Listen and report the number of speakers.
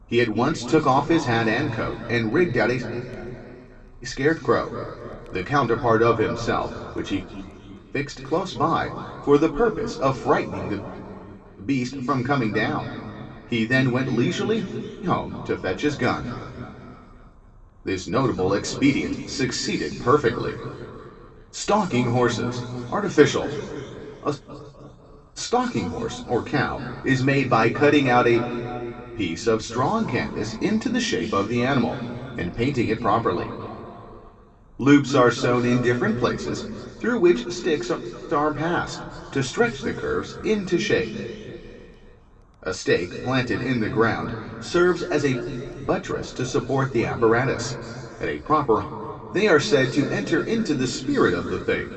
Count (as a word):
one